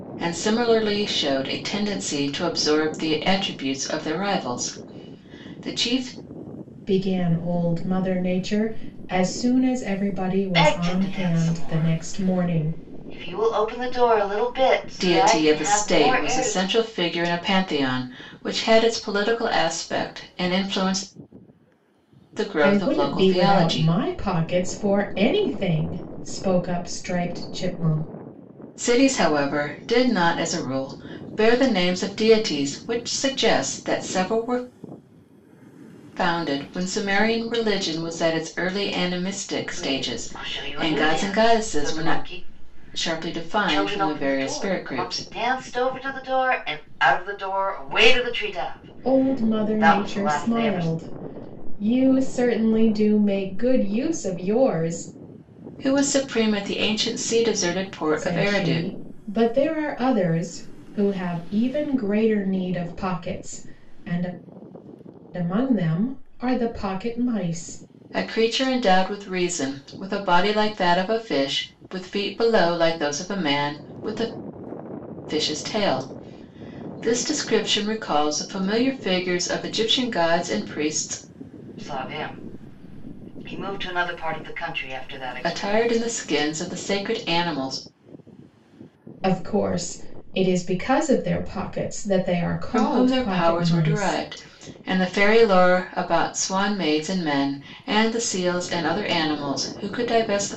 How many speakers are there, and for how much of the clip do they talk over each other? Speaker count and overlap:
3, about 15%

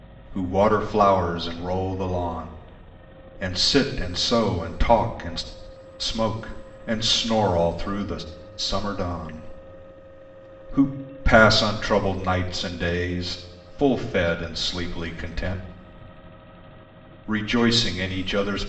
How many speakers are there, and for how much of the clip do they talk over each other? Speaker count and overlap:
1, no overlap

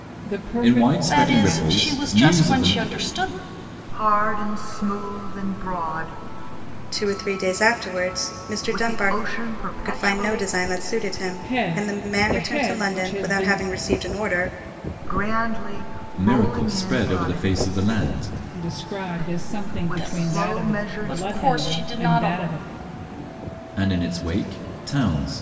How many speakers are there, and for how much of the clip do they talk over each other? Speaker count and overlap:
5, about 40%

